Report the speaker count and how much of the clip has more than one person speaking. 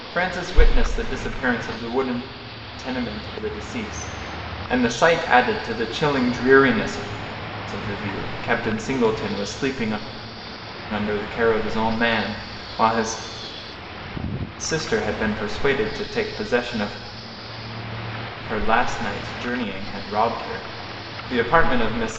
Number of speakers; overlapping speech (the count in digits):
1, no overlap